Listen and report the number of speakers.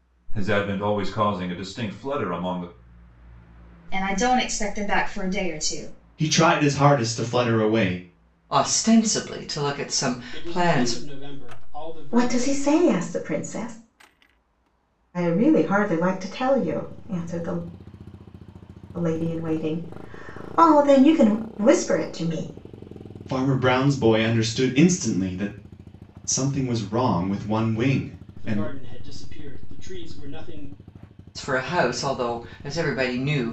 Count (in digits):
6